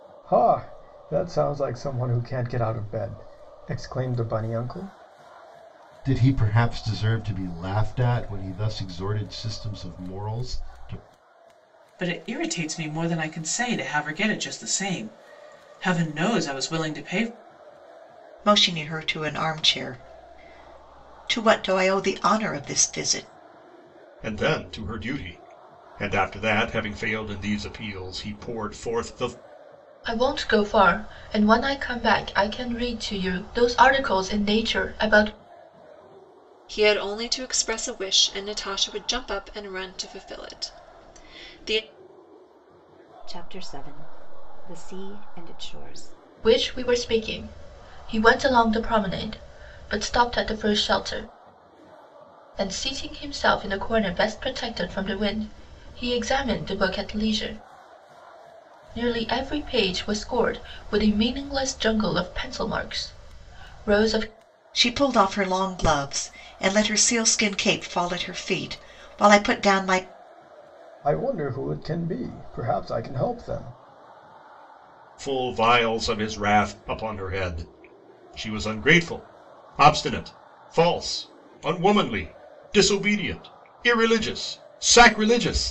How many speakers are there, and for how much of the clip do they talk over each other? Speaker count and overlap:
eight, no overlap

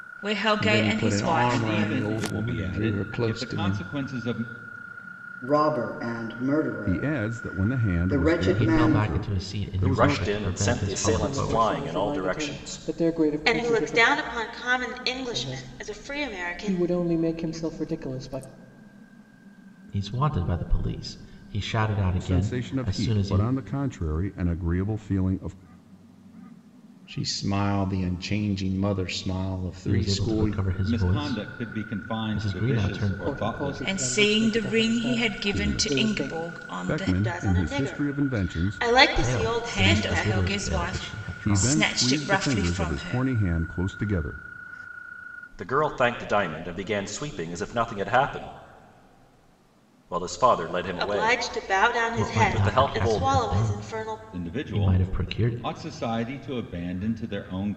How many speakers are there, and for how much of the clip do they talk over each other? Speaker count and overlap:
nine, about 53%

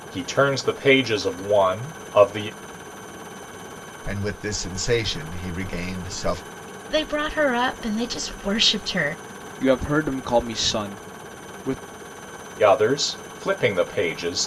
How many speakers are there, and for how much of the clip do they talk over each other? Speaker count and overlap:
four, no overlap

